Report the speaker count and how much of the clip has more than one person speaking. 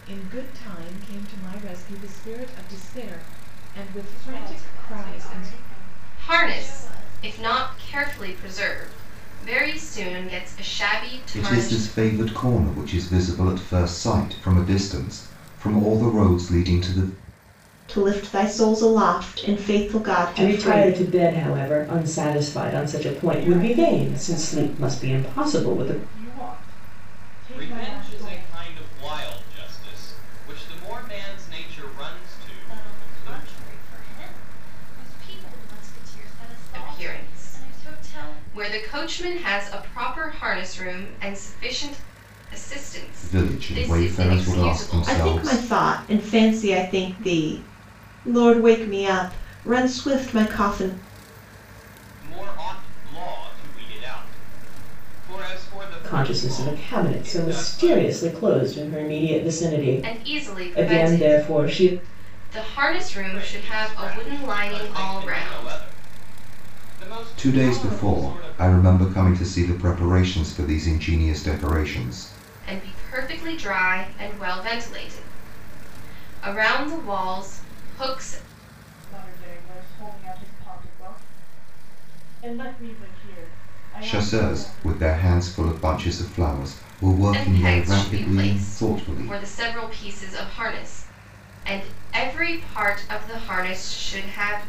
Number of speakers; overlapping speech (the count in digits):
8, about 25%